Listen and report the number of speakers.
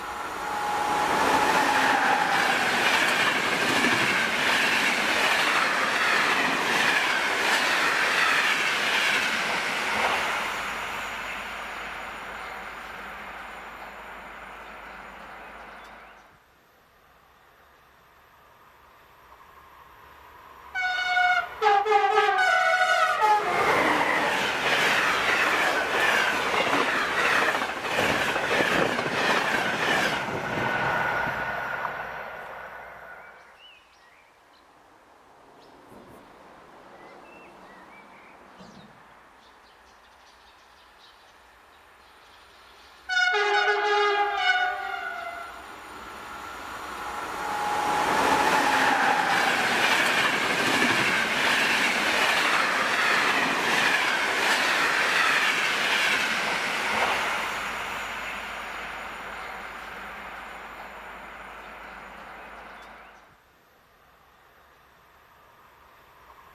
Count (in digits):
0